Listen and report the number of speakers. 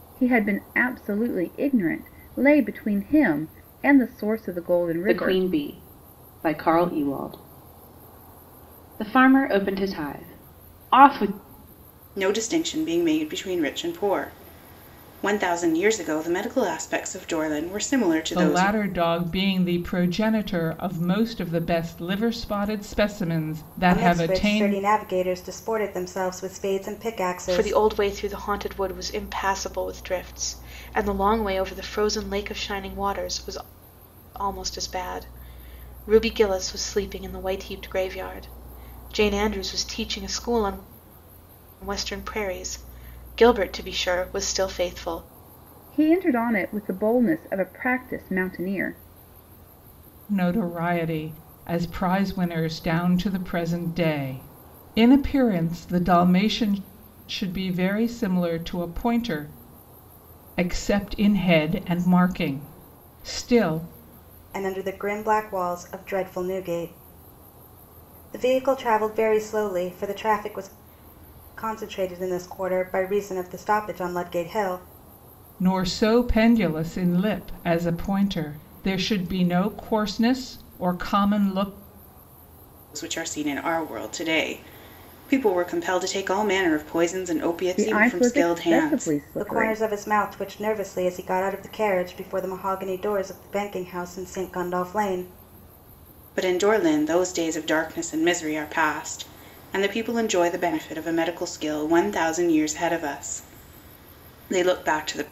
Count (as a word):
six